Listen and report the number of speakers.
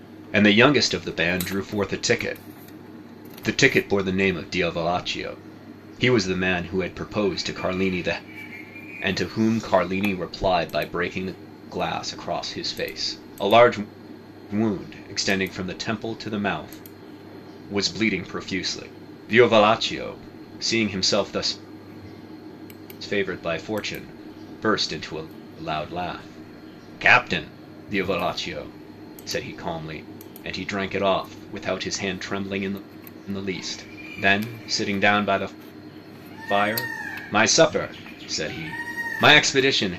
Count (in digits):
1